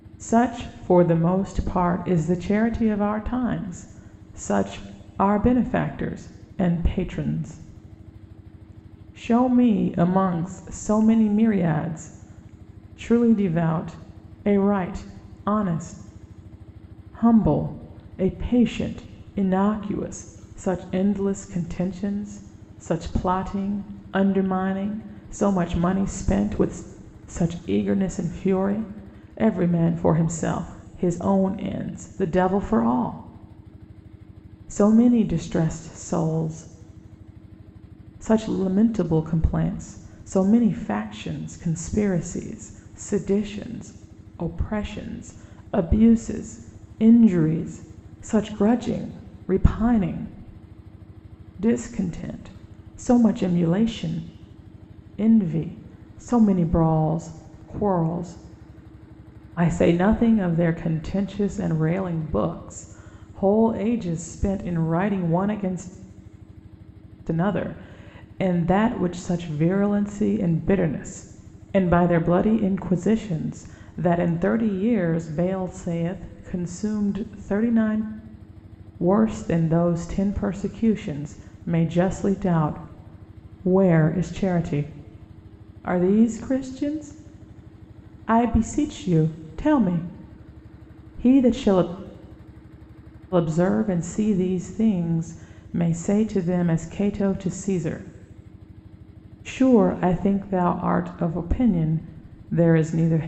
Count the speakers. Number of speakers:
one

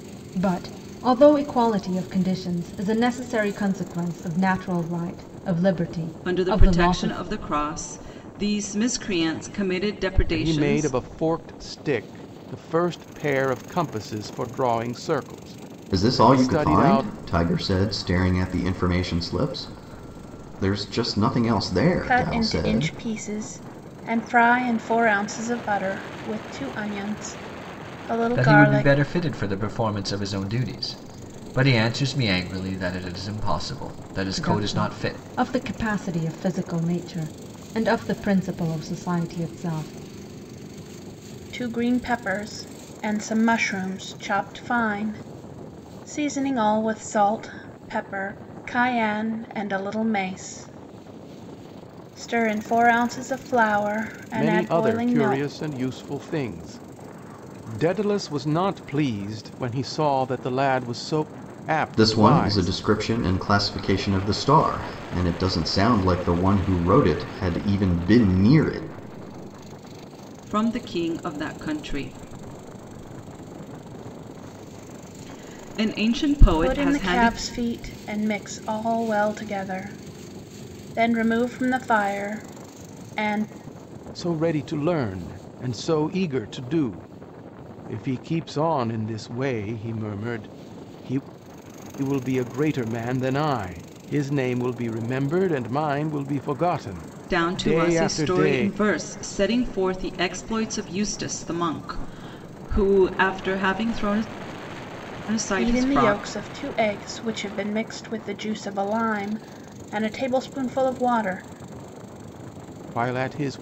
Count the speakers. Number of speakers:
six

